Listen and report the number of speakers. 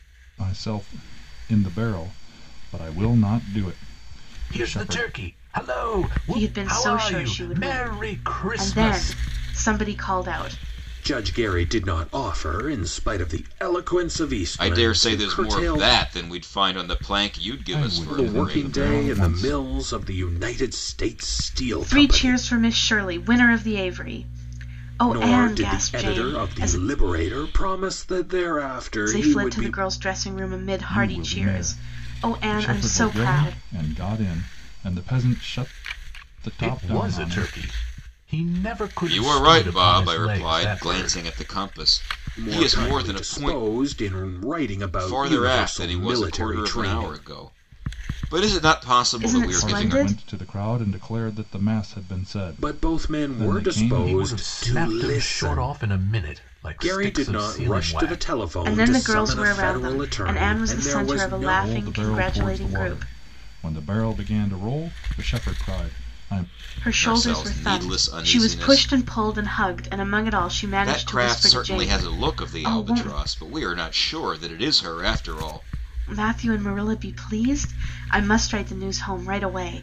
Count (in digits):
5